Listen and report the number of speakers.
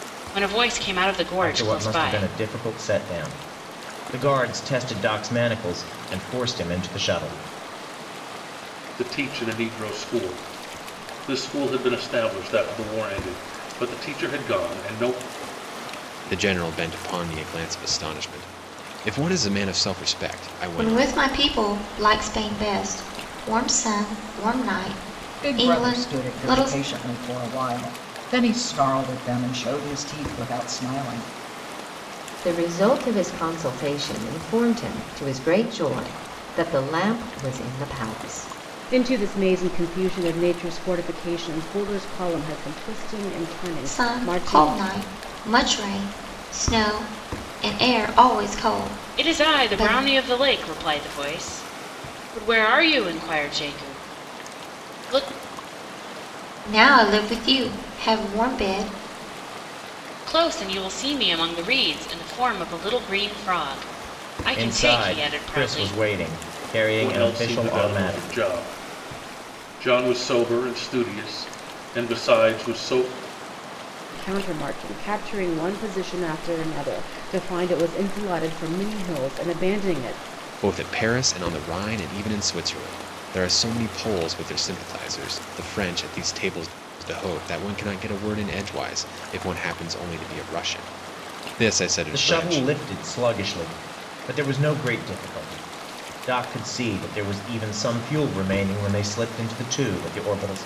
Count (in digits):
8